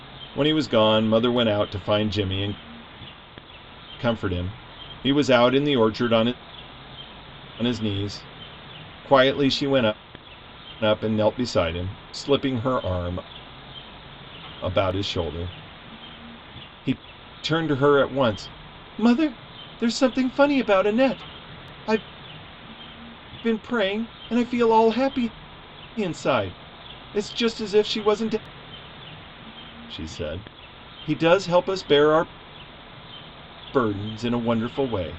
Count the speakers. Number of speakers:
one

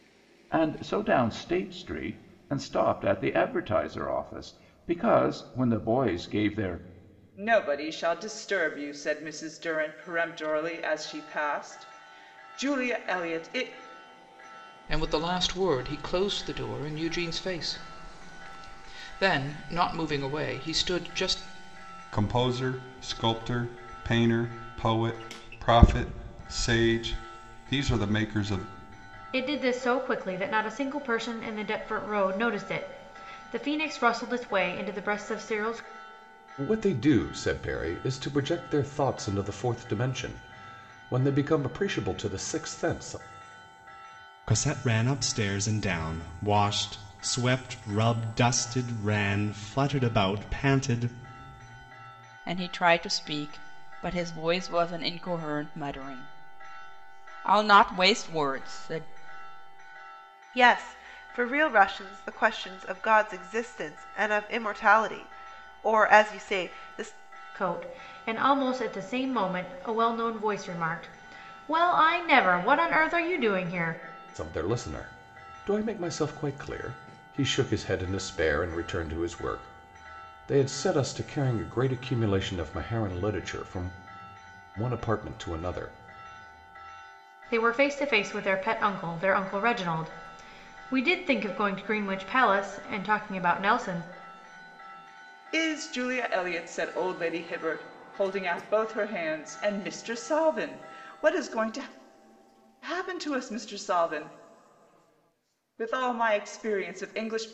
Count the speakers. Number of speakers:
nine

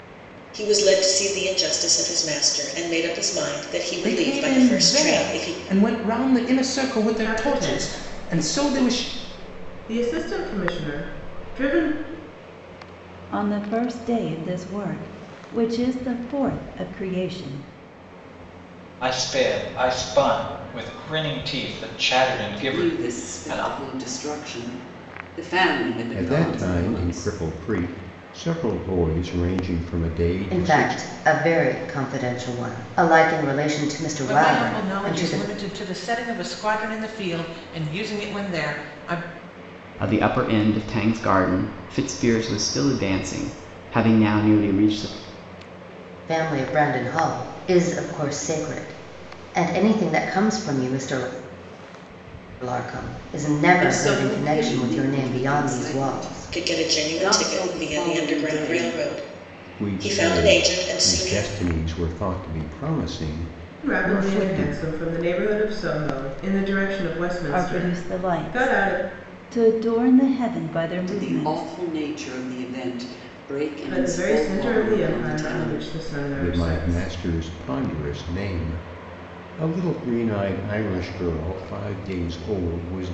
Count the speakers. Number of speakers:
ten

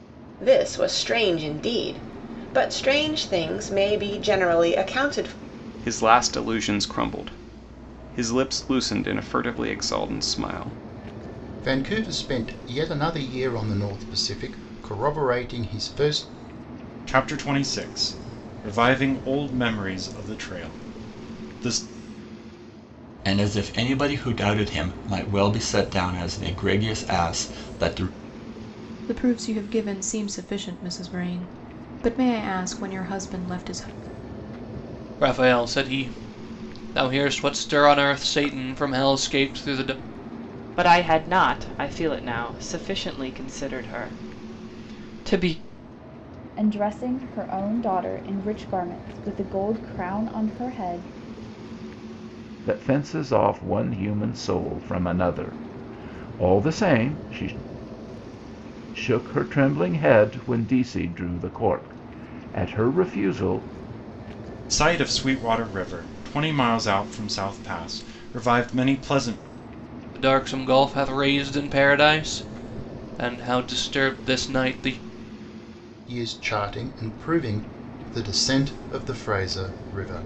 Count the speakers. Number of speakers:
ten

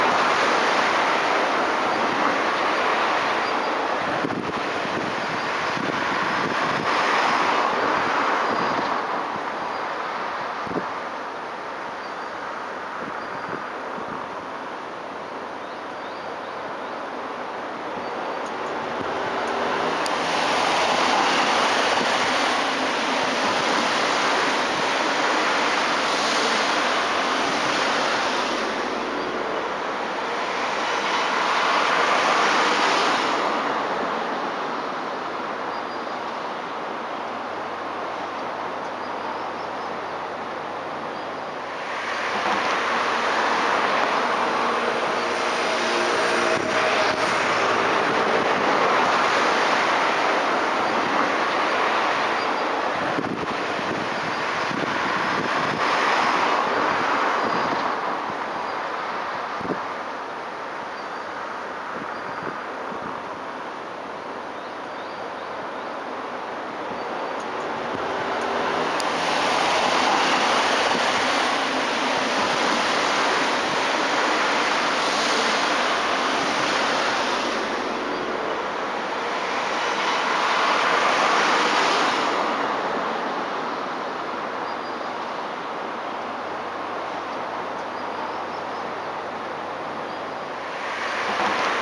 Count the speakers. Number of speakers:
zero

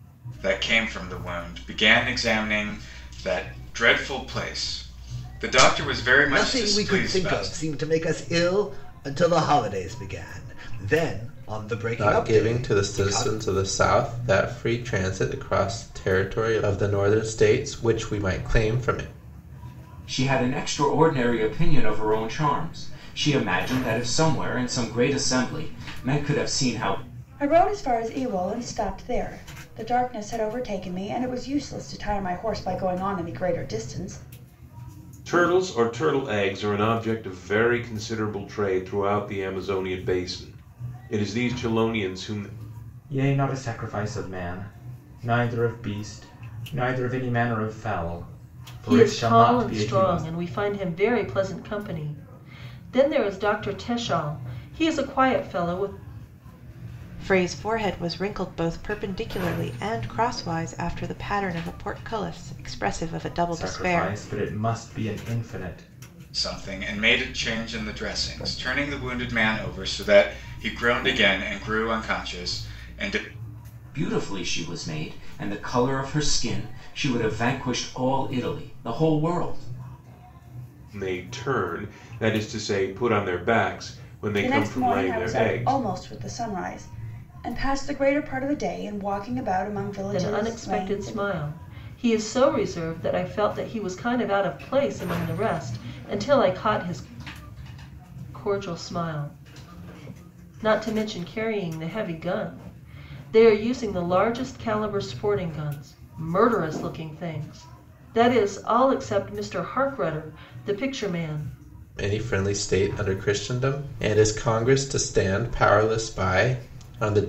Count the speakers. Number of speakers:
nine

